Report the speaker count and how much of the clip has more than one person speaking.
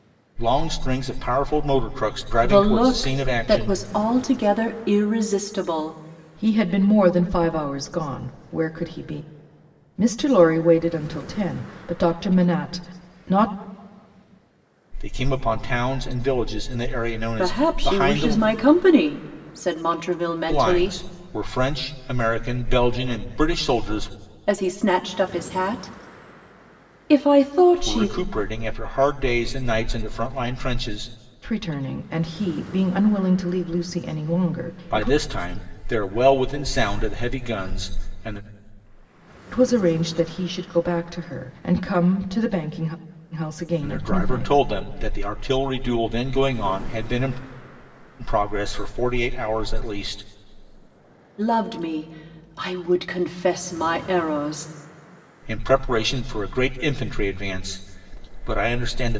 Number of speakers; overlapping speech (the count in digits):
3, about 7%